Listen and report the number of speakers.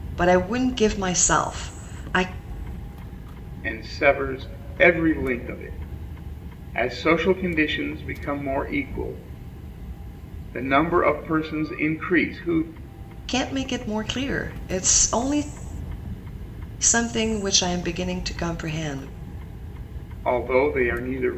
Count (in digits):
2